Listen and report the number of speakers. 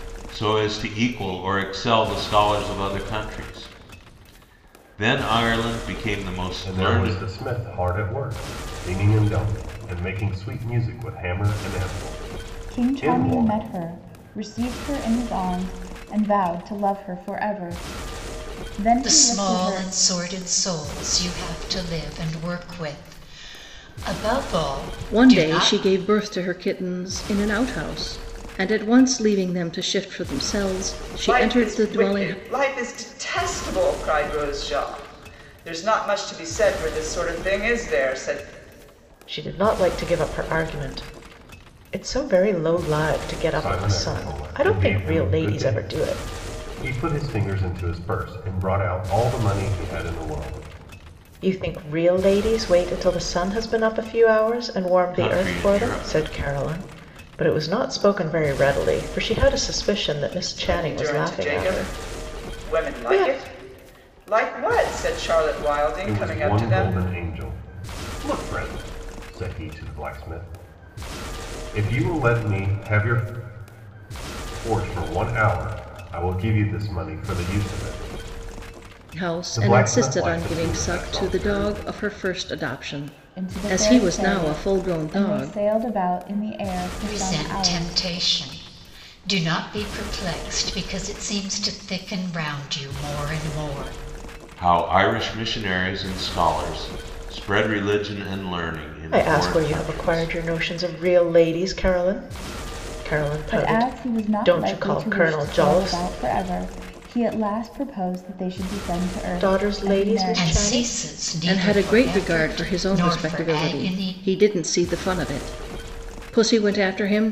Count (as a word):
seven